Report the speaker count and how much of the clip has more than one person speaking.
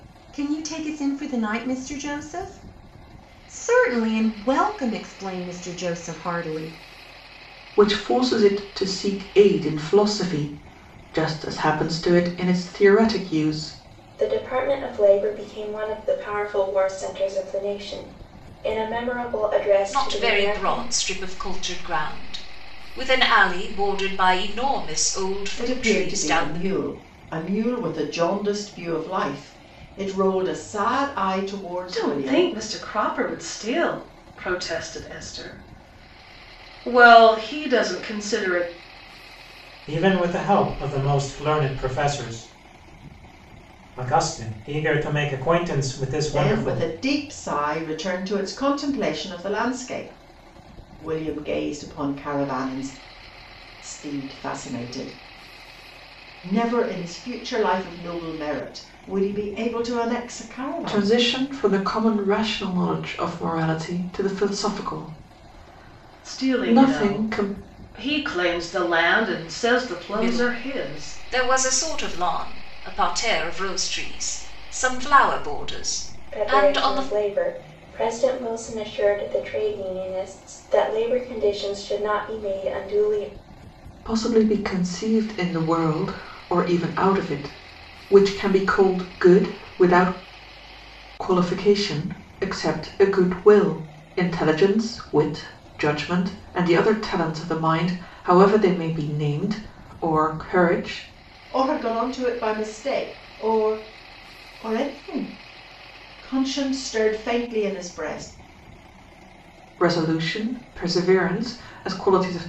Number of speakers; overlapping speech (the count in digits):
7, about 6%